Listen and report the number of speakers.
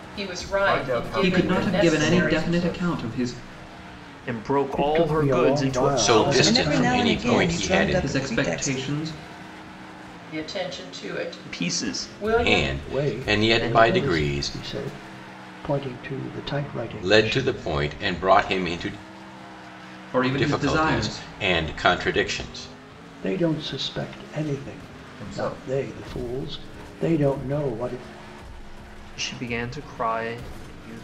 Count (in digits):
7